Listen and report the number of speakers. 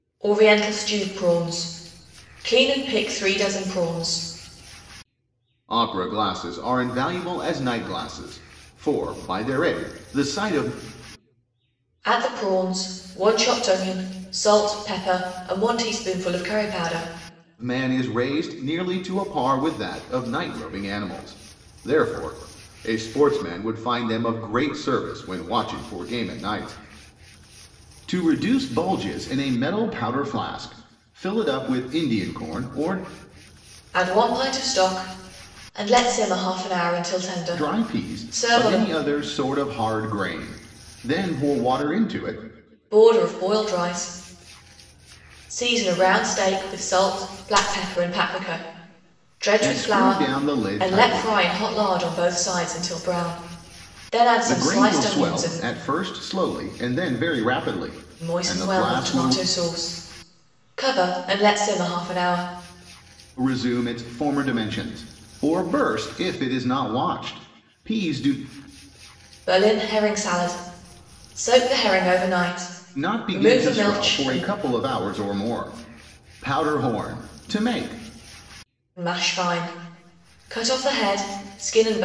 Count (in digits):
2